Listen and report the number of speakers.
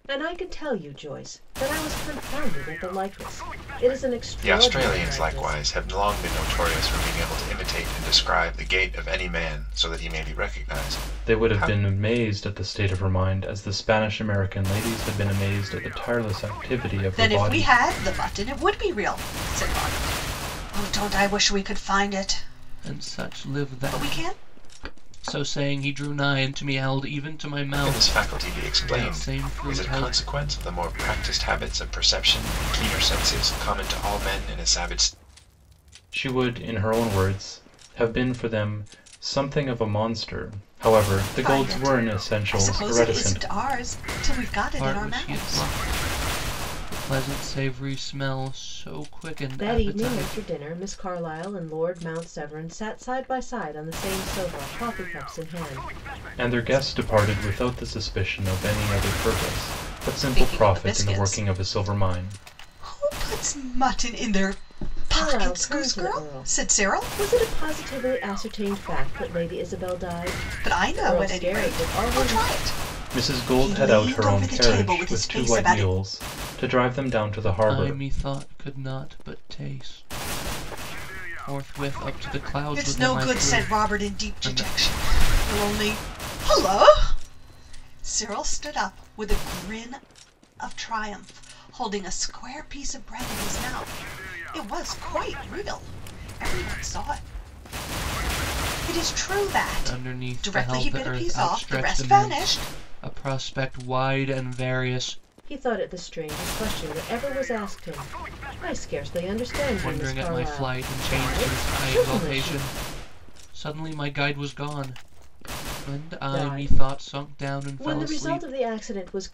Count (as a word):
five